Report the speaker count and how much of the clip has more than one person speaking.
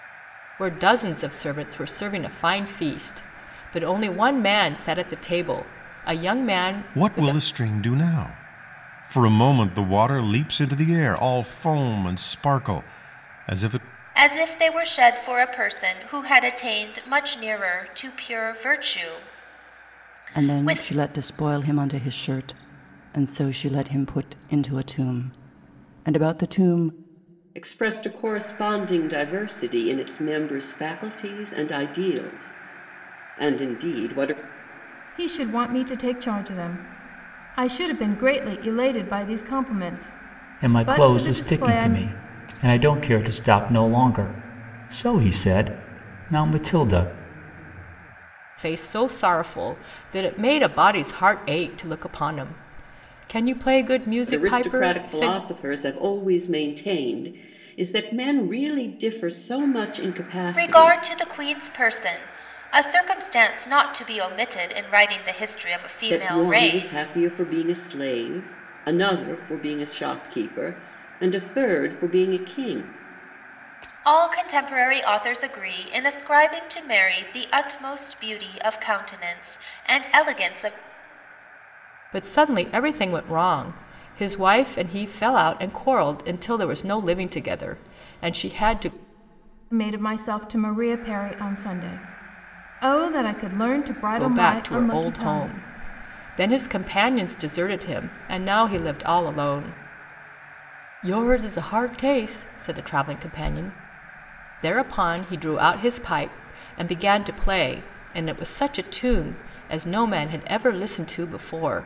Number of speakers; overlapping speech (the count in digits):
7, about 6%